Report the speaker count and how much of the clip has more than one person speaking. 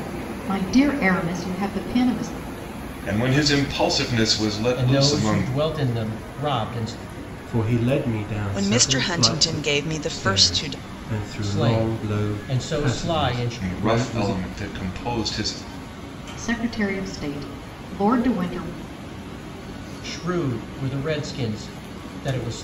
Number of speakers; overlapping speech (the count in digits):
5, about 25%